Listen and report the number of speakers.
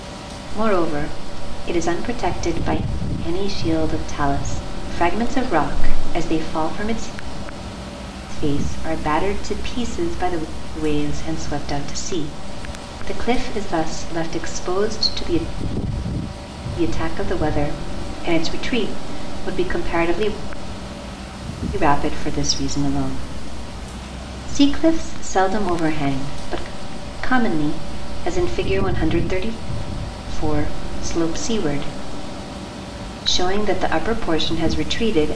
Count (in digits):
1